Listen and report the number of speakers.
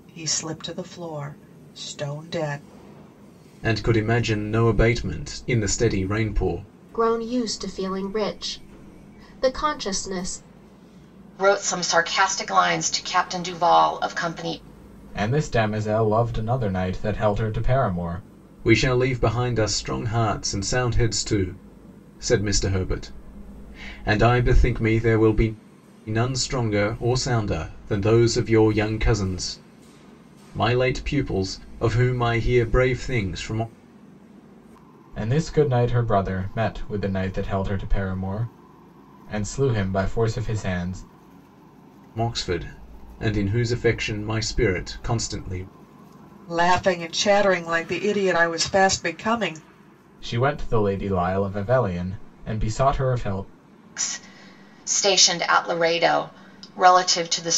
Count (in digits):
5